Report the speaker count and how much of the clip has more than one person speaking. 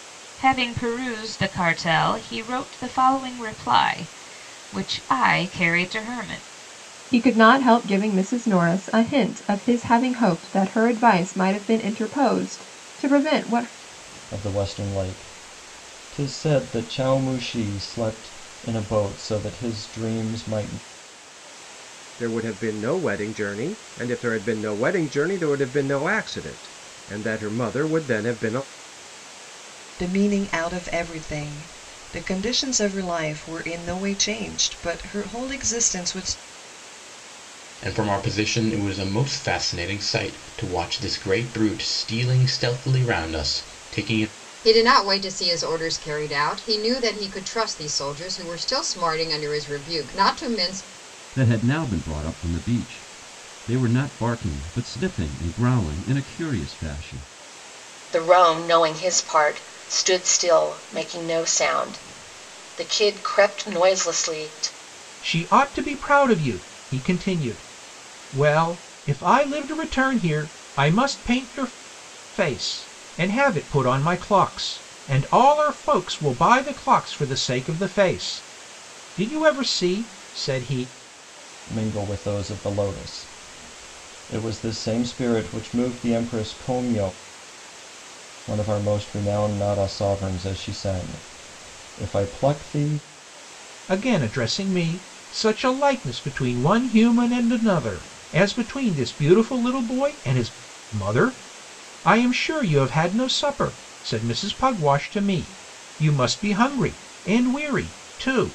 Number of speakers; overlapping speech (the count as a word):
ten, no overlap